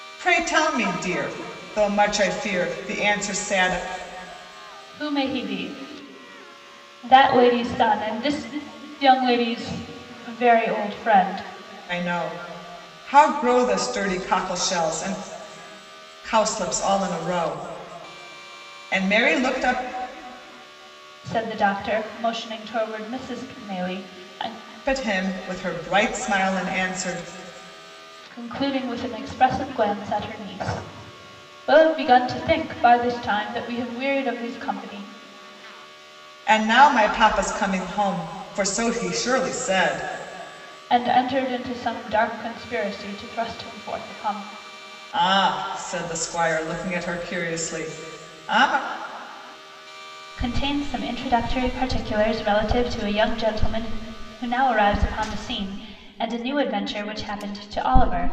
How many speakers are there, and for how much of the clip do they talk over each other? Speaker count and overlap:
2, no overlap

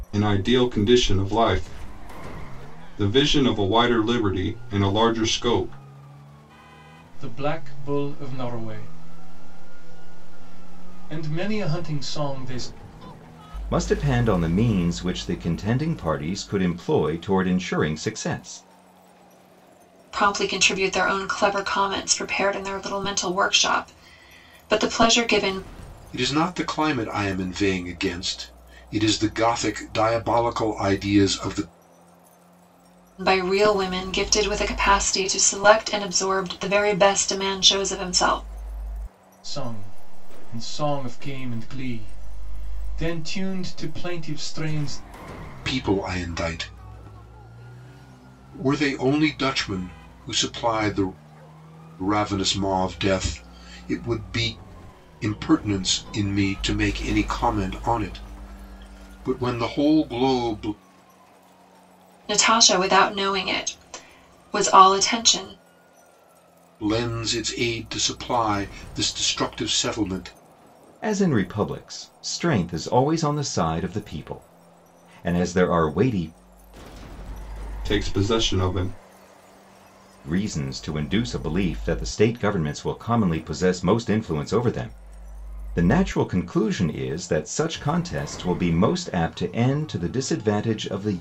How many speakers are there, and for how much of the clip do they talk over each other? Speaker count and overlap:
5, no overlap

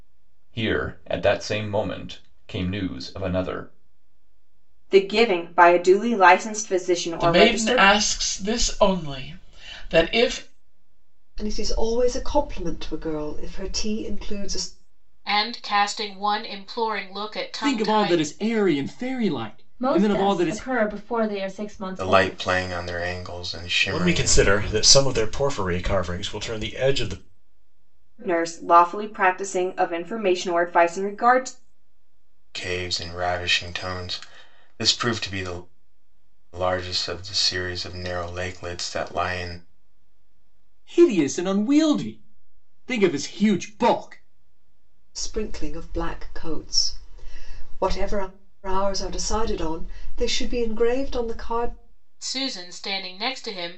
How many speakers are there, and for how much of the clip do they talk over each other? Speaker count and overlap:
9, about 8%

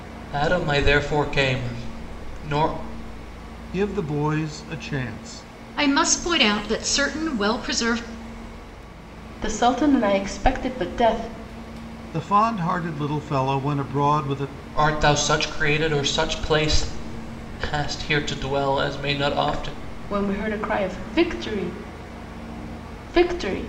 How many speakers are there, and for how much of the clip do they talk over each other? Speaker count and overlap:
4, no overlap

